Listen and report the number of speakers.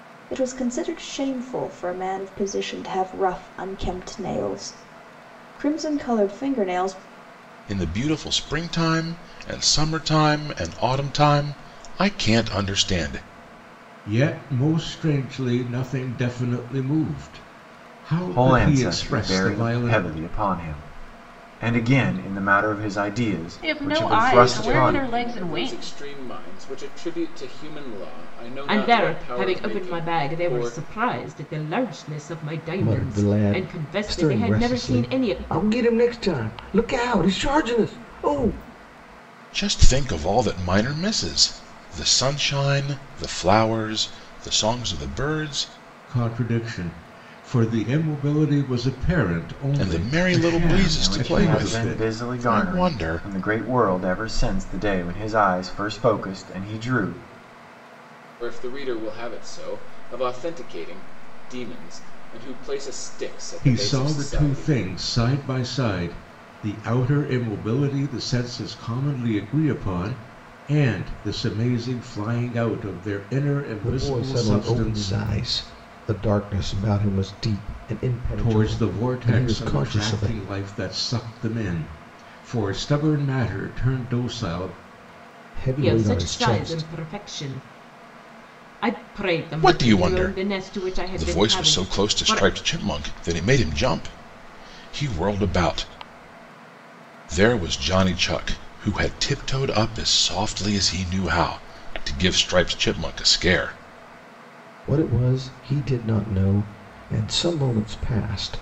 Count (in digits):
8